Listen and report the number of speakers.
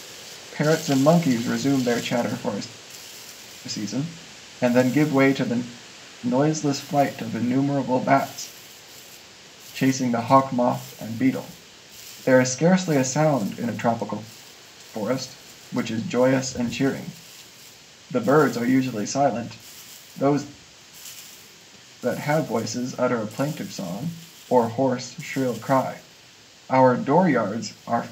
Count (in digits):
1